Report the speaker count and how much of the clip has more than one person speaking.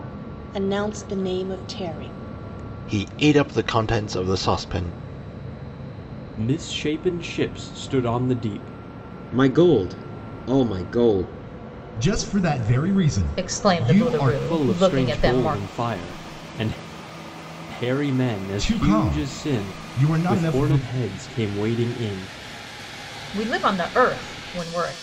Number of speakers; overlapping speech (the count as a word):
six, about 17%